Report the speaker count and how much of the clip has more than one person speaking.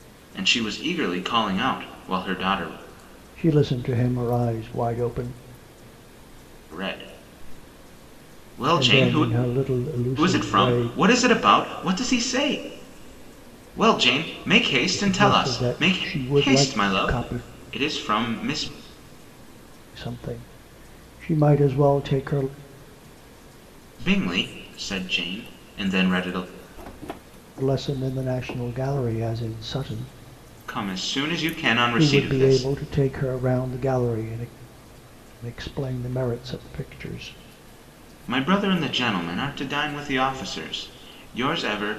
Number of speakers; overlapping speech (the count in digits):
2, about 10%